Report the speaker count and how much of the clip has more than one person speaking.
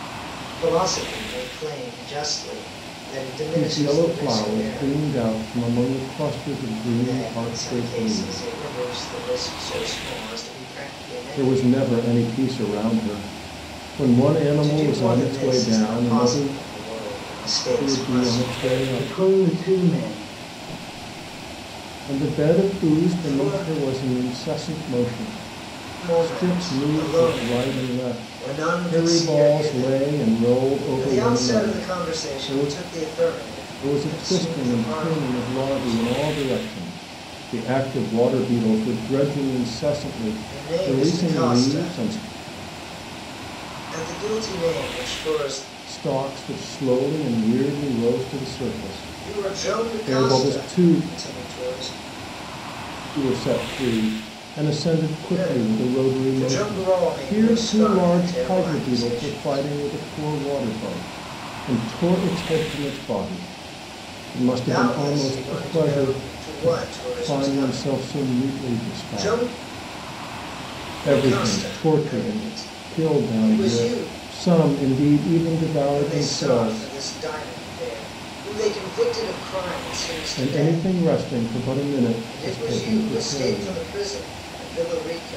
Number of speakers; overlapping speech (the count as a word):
two, about 41%